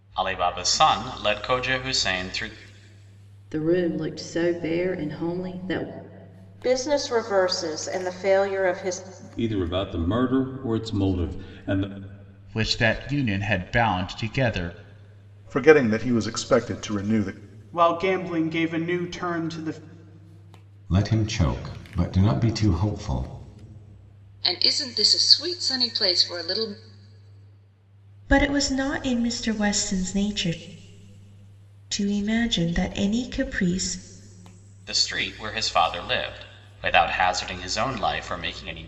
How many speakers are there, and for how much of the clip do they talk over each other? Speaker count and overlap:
10, no overlap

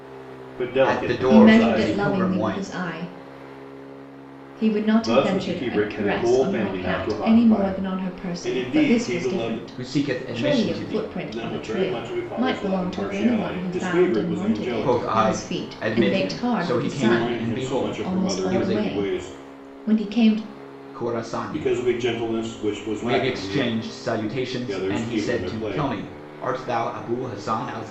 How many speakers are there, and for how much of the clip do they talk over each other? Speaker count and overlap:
3, about 69%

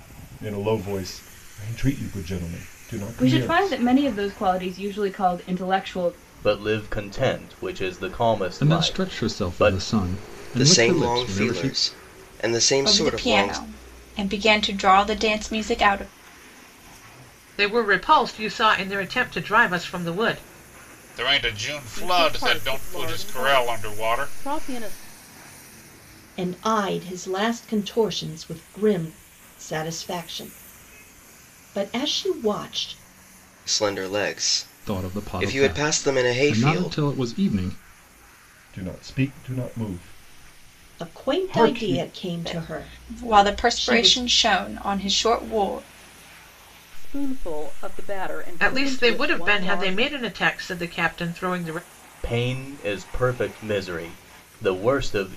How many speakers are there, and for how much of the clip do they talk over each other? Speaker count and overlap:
10, about 24%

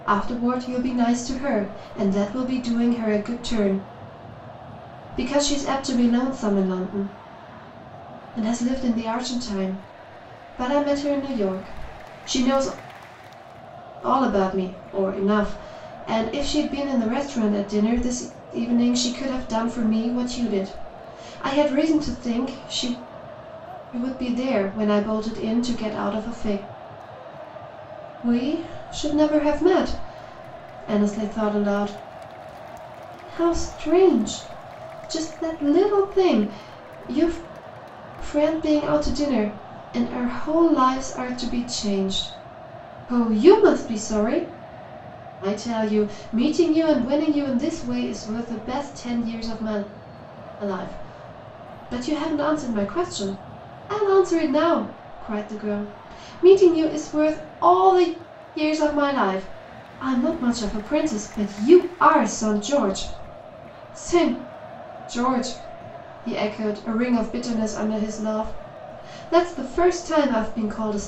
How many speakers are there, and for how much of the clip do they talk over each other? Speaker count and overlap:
1, no overlap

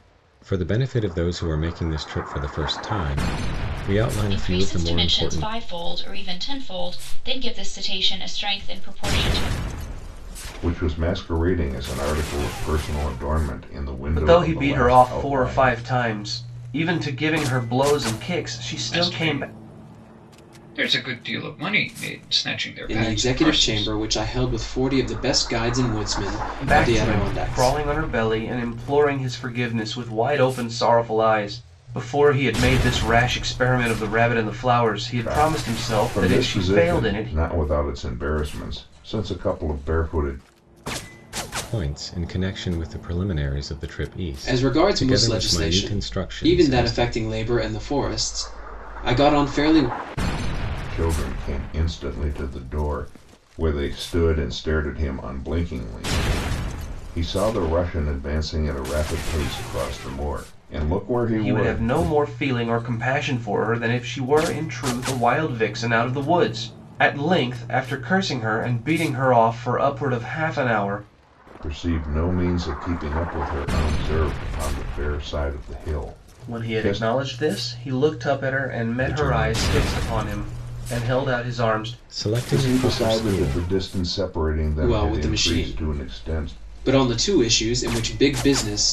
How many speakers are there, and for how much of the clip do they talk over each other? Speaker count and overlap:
6, about 20%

